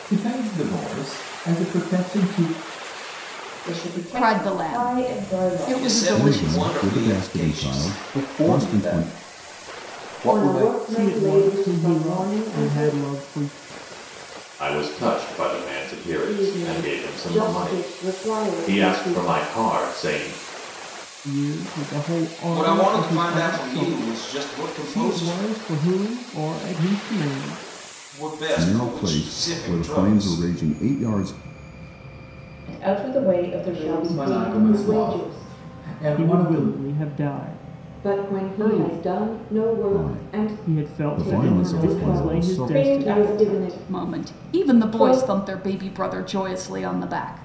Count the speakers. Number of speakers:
9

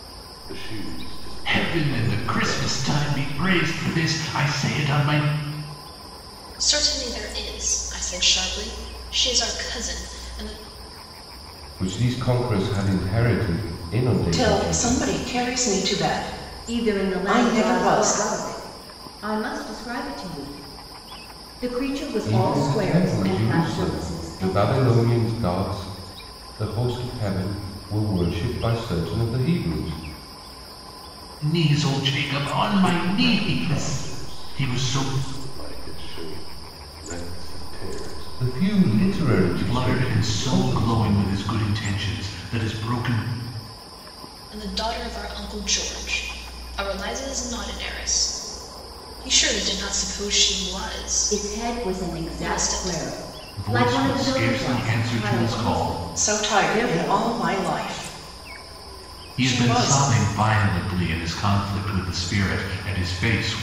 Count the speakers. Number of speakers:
6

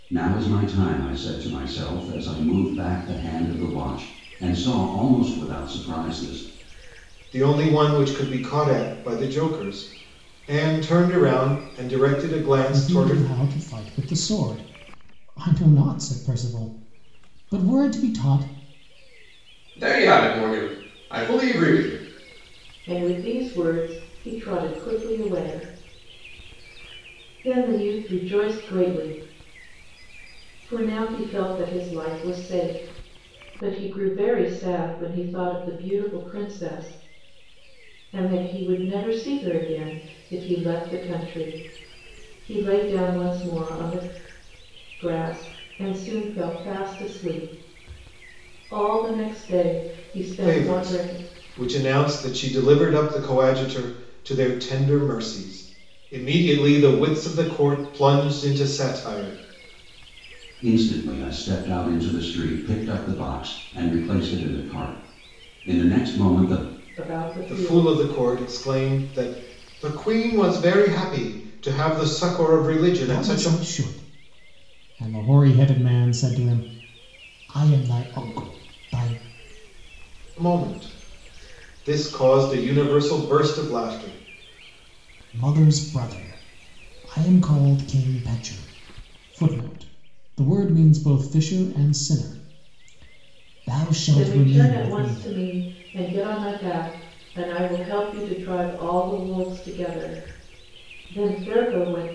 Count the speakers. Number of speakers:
5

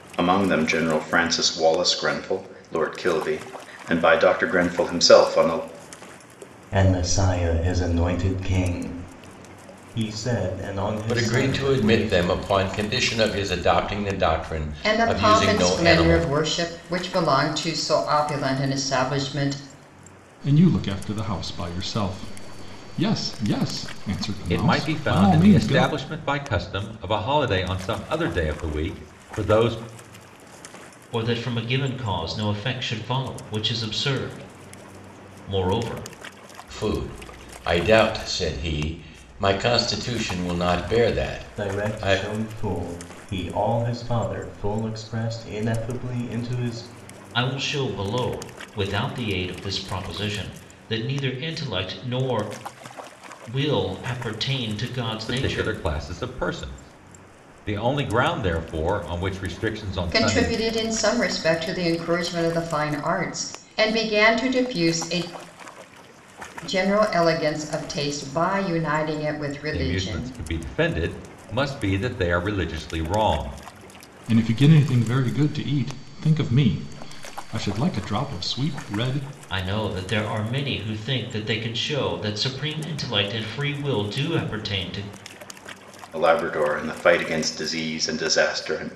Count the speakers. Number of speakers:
7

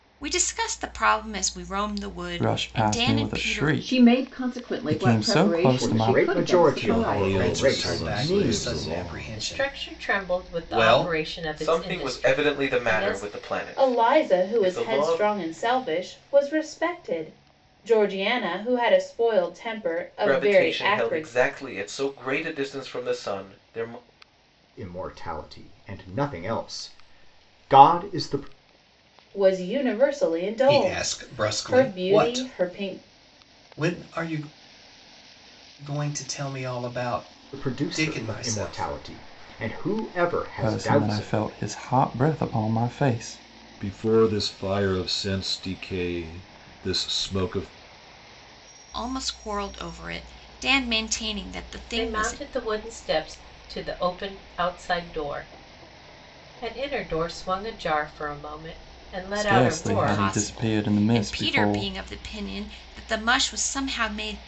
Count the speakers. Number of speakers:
9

